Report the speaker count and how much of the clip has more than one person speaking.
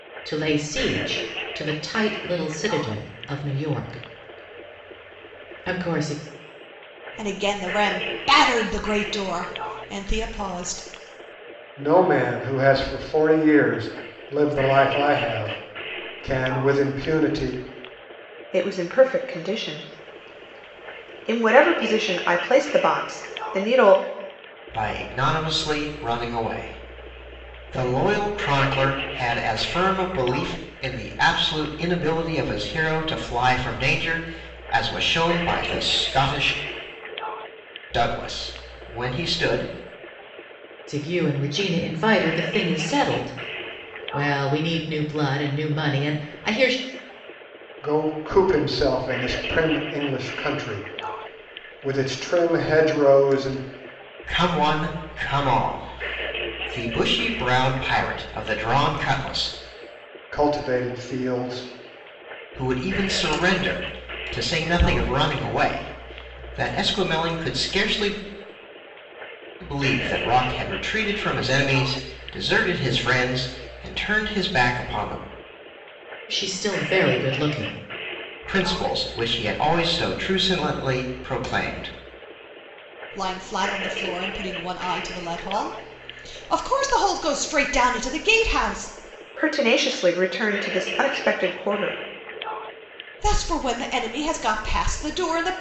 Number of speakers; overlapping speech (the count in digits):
5, no overlap